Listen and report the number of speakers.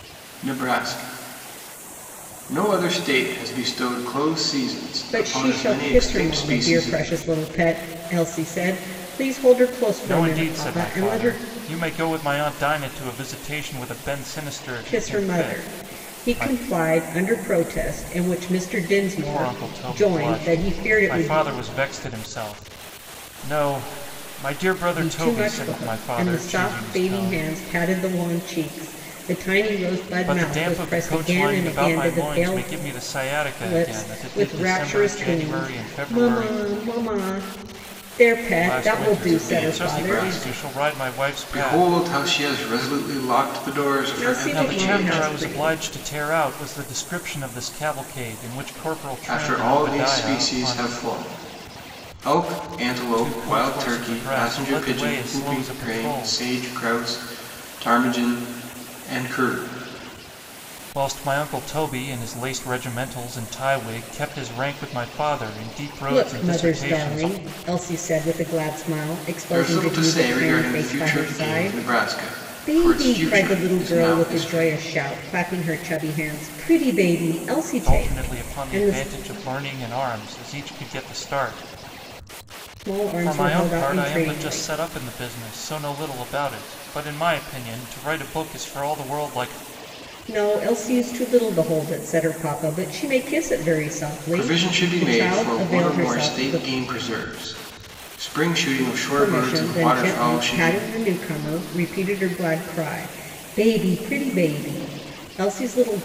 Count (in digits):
3